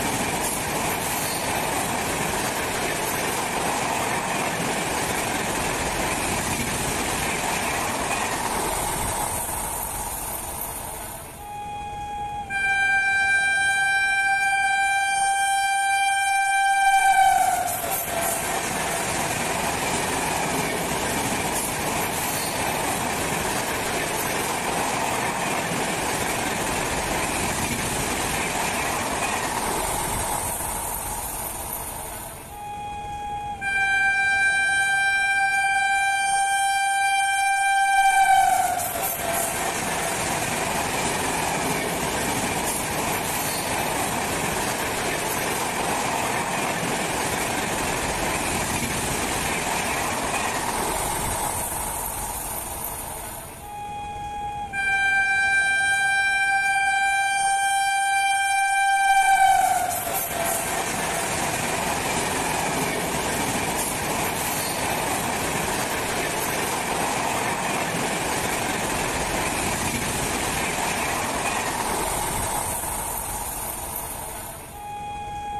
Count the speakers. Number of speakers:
zero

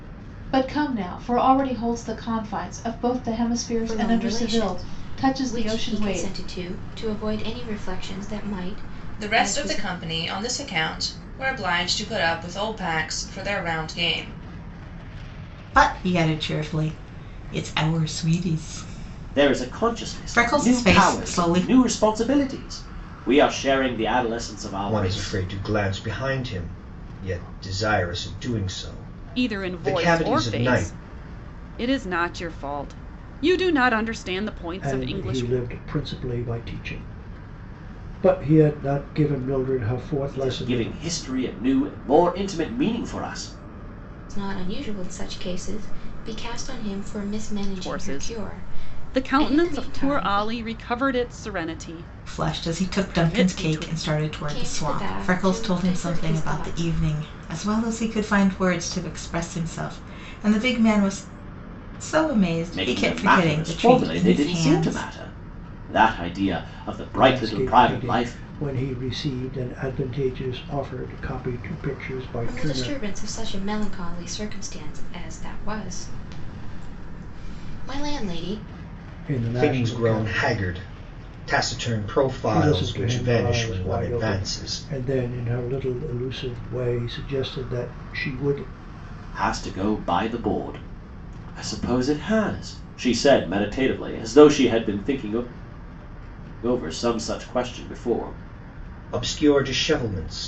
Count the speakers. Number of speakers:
eight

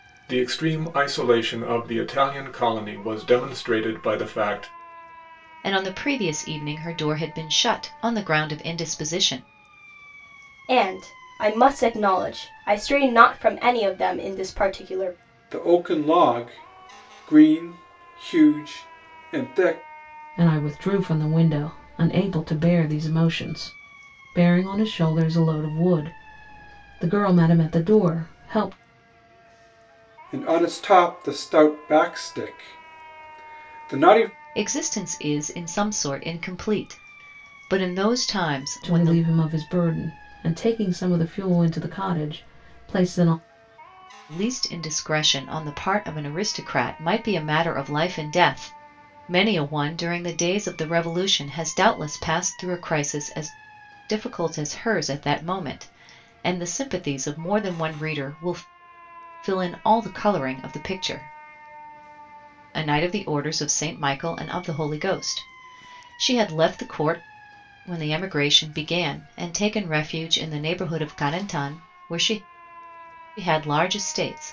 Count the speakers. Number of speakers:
five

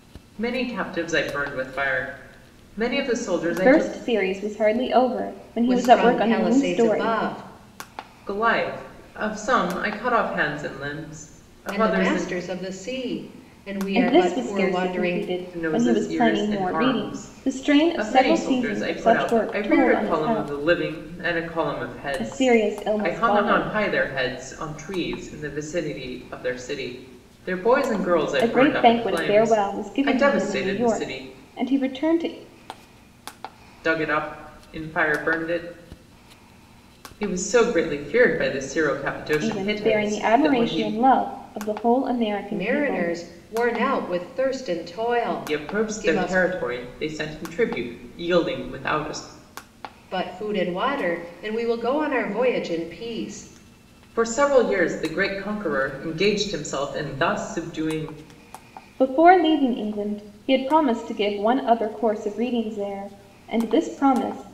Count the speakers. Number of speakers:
three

